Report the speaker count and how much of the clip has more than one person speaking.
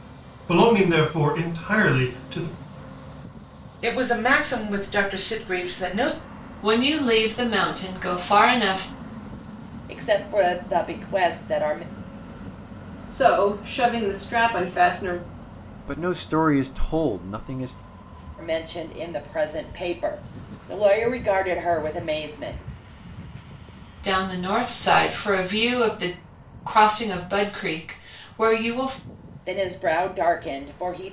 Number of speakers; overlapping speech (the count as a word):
six, no overlap